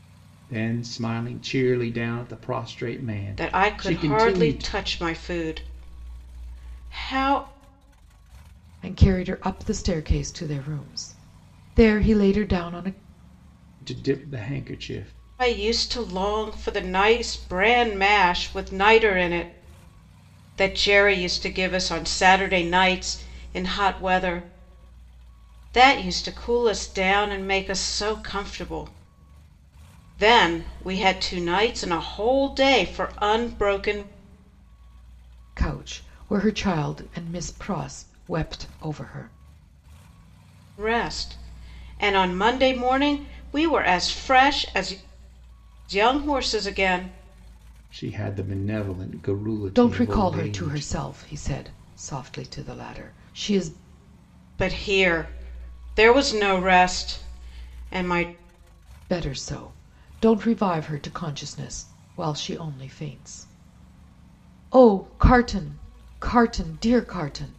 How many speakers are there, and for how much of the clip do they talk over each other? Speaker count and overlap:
three, about 4%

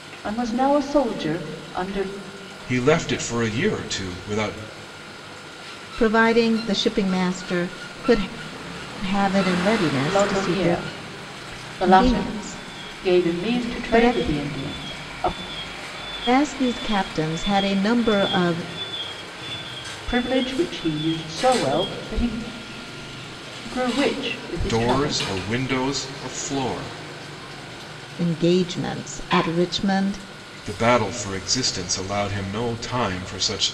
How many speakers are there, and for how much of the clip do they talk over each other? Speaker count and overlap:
three, about 10%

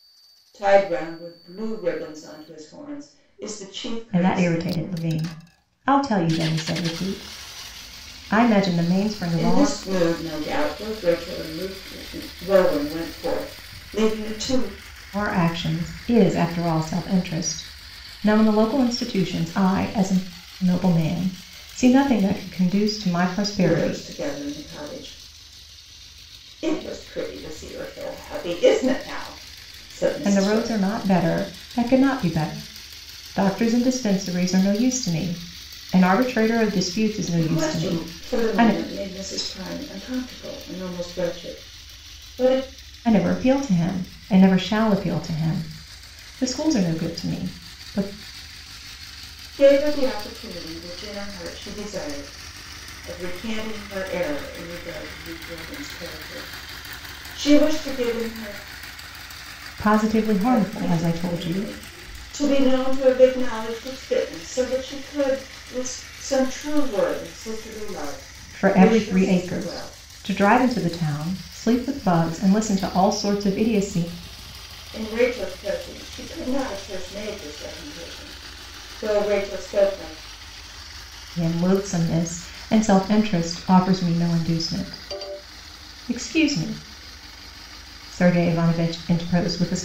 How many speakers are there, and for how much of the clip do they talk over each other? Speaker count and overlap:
two, about 8%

